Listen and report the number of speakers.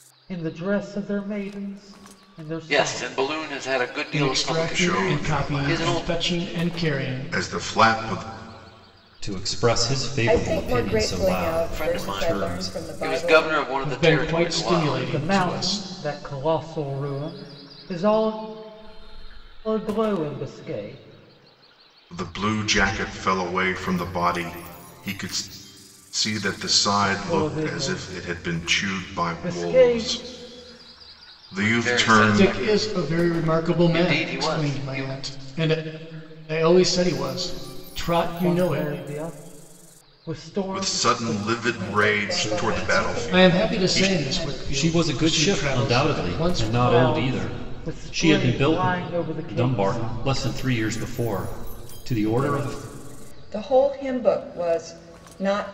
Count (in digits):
6